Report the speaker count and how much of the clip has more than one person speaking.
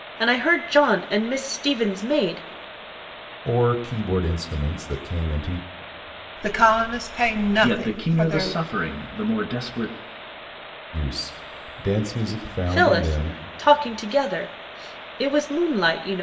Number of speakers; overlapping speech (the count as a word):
four, about 10%